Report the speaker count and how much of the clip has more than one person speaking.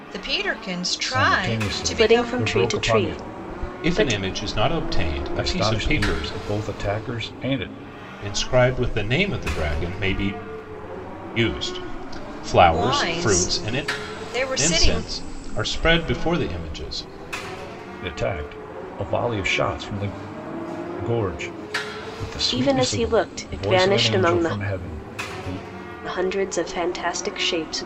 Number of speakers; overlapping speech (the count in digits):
4, about 25%